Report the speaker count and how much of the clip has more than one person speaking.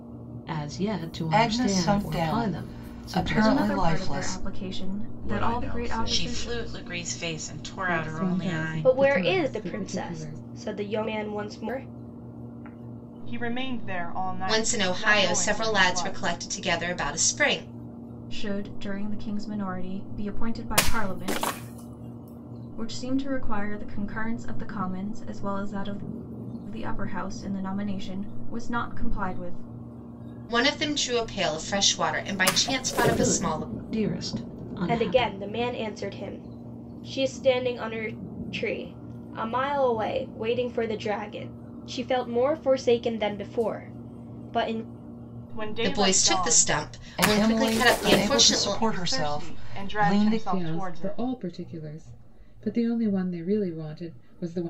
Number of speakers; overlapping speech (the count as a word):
nine, about 28%